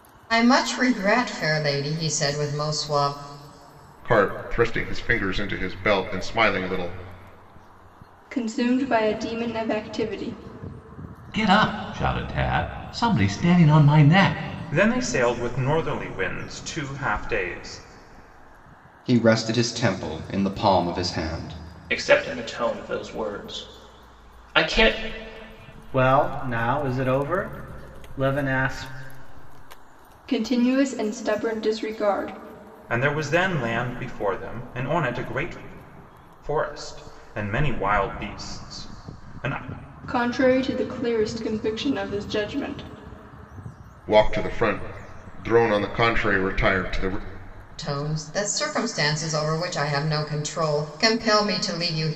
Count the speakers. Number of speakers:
8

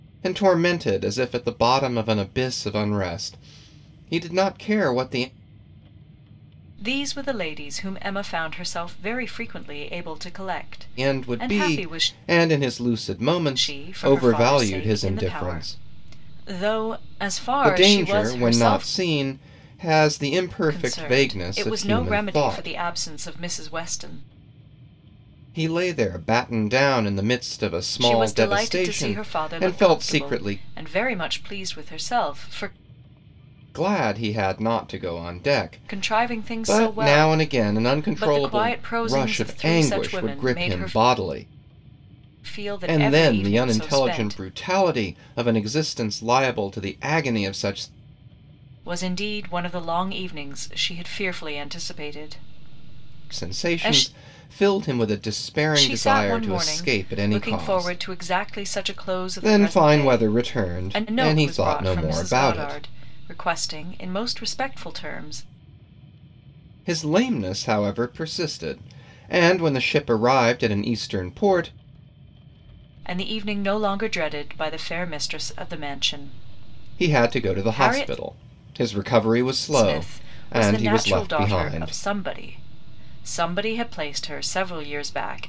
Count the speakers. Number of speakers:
2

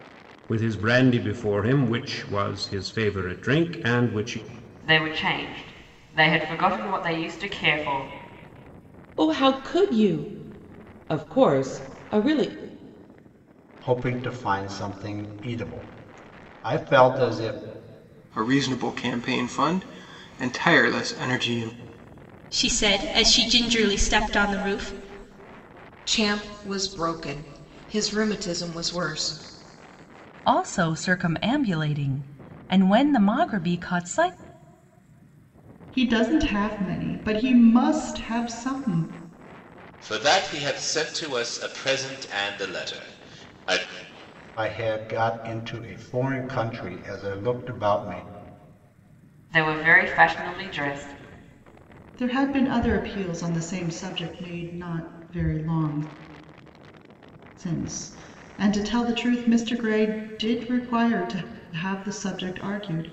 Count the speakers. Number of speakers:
10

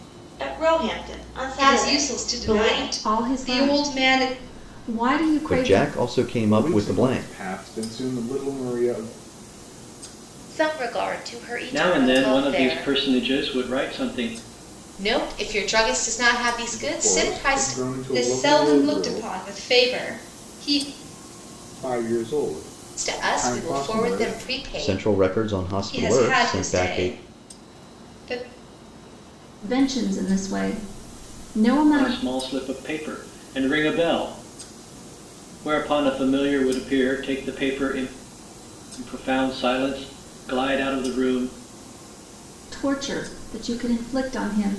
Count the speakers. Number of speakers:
8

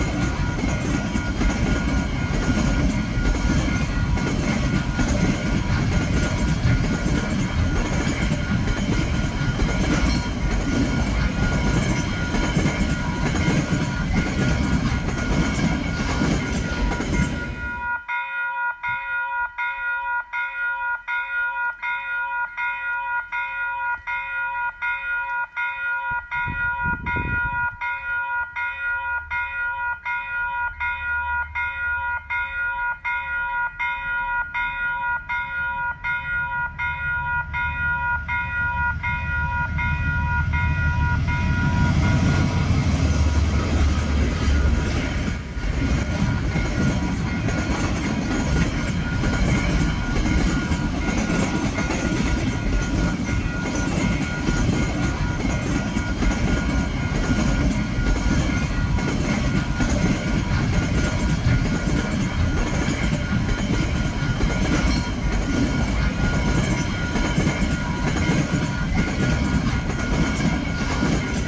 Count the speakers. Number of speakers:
0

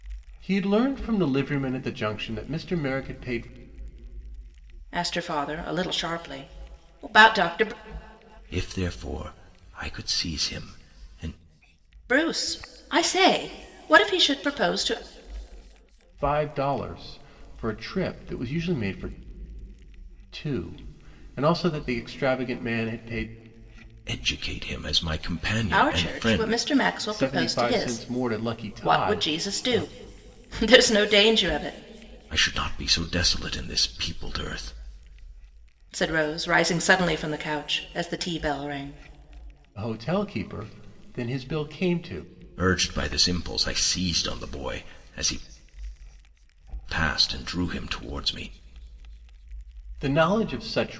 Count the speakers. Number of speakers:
3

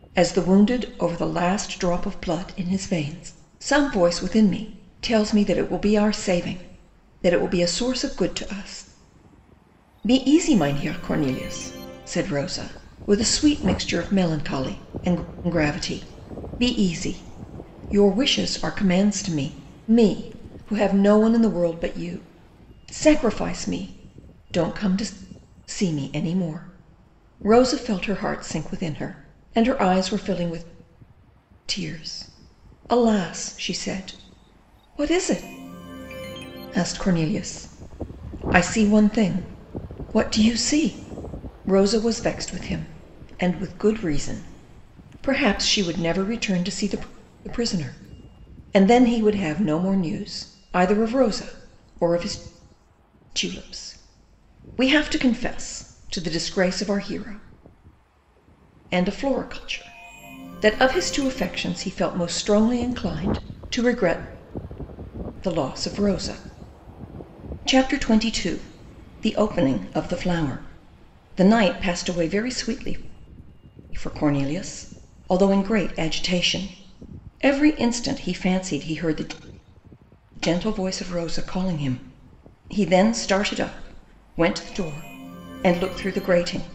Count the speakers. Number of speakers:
1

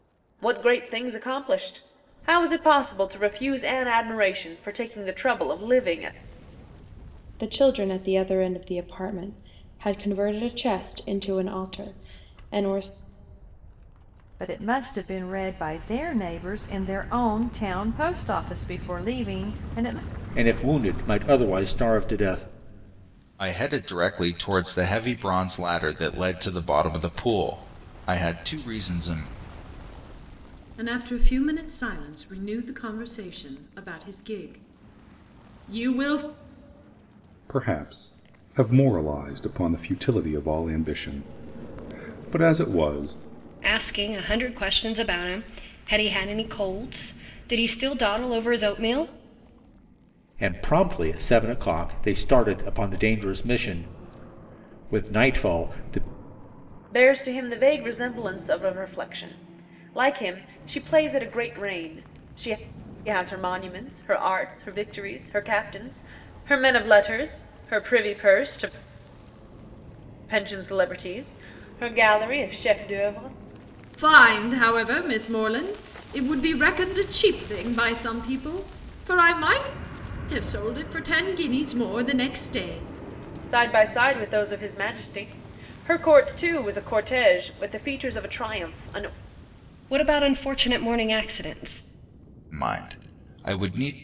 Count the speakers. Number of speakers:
8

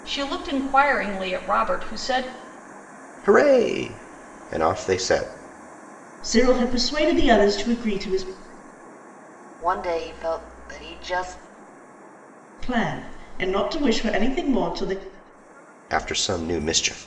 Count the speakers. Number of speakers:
4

